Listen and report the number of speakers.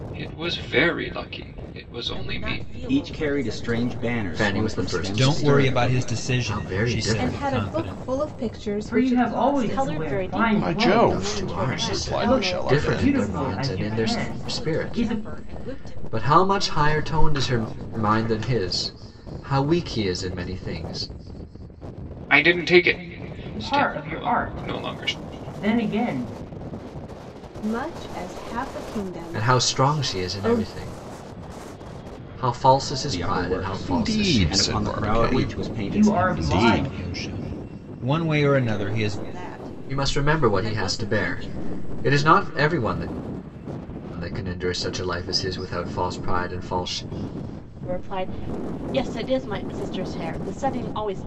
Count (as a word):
nine